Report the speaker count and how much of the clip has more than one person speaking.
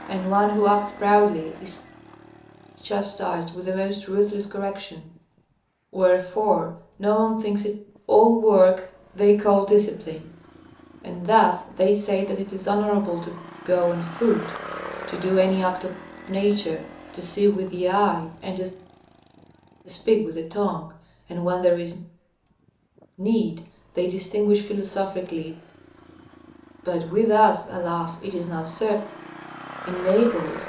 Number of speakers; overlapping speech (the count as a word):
one, no overlap